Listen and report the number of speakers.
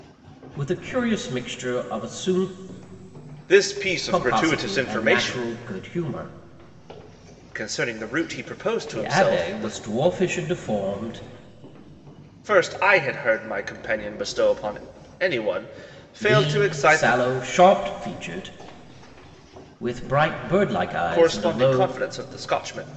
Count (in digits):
2